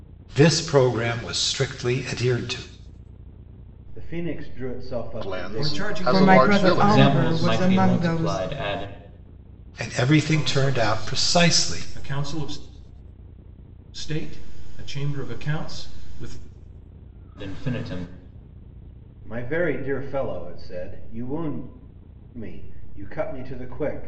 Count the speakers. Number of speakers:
six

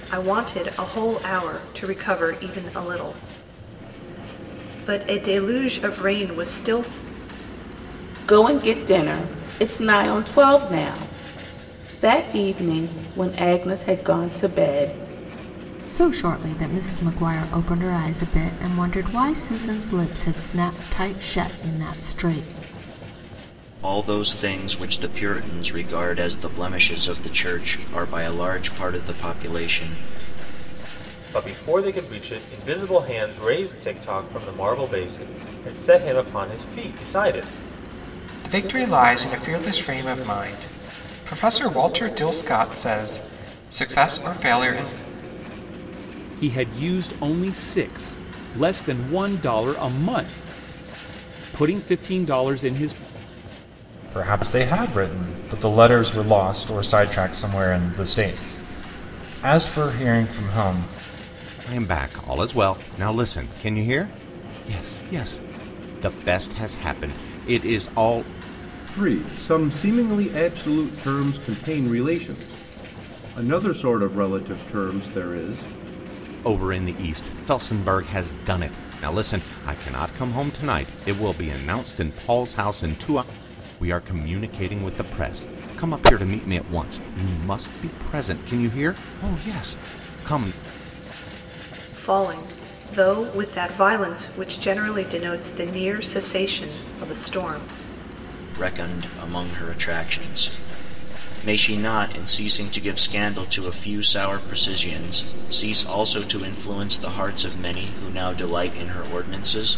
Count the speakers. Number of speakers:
ten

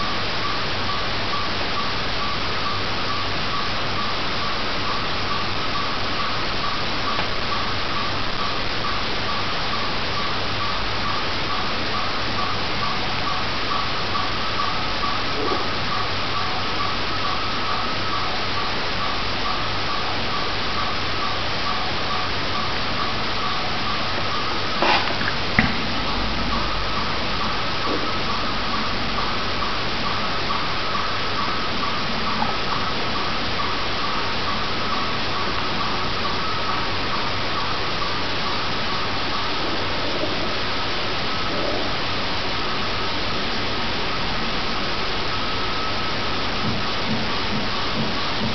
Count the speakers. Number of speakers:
zero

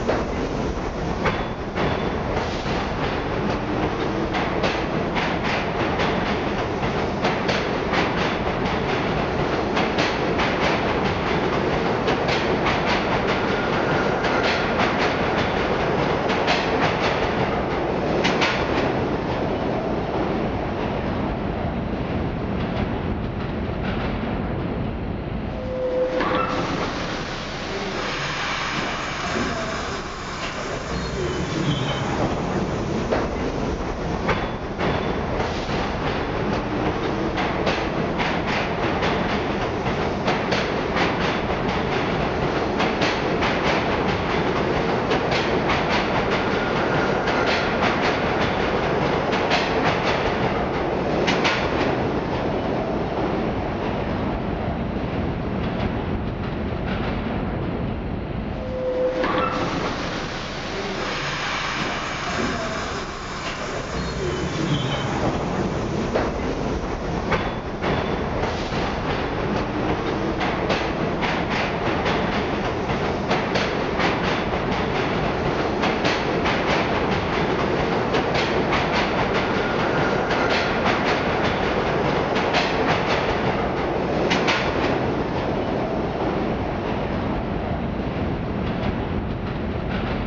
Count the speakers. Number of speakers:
zero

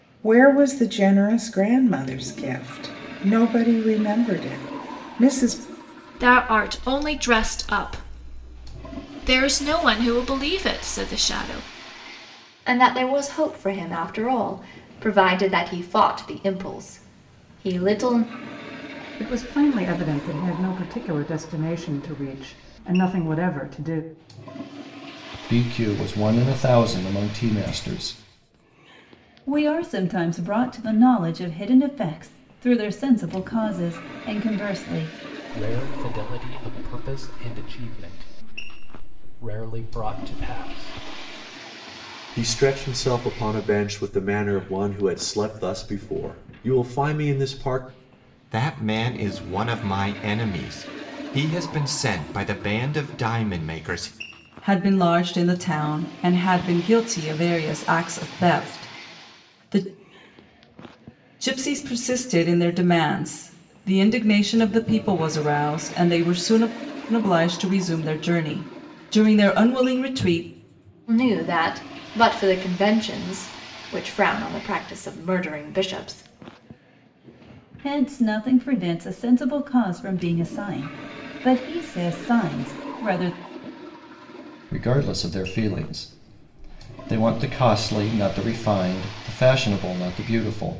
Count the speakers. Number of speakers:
ten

